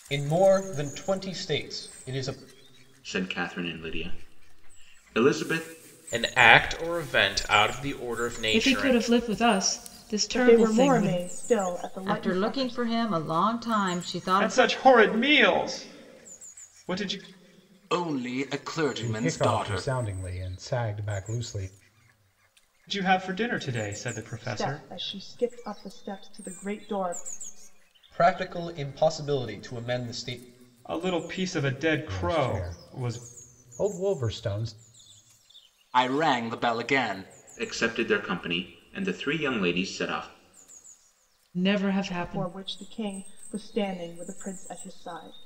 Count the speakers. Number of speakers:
9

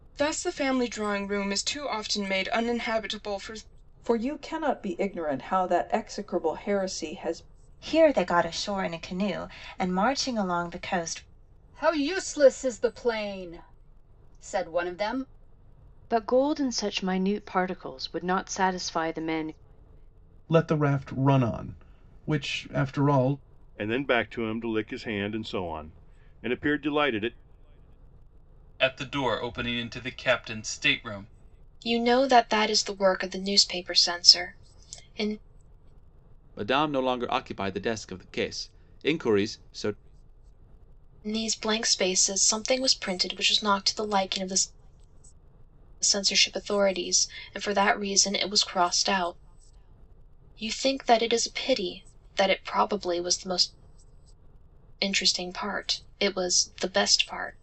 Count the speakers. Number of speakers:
10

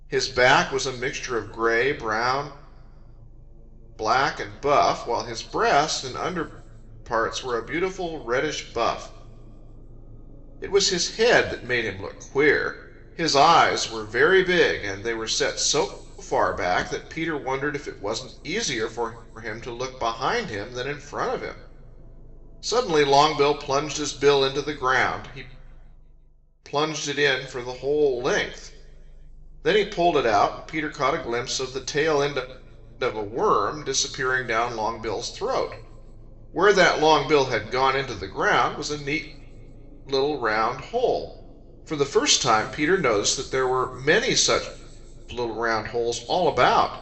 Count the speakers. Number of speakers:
1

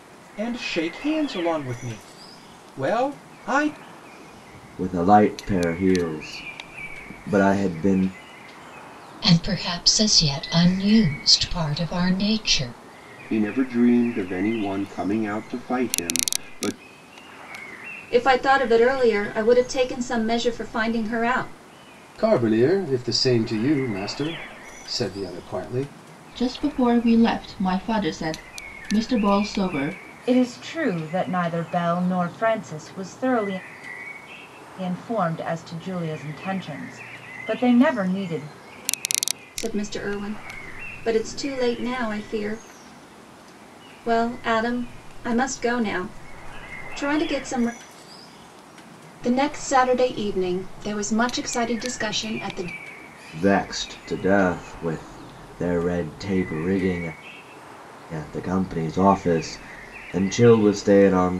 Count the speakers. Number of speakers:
8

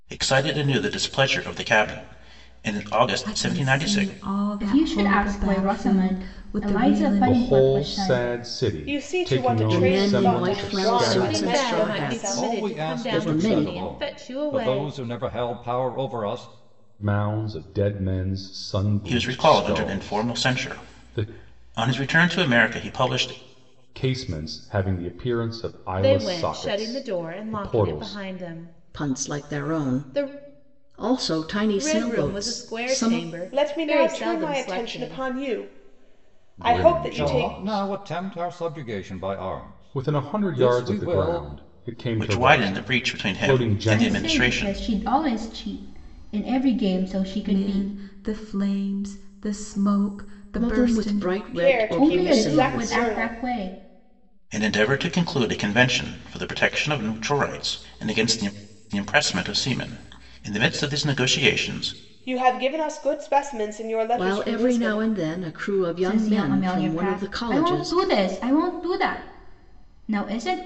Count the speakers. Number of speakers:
8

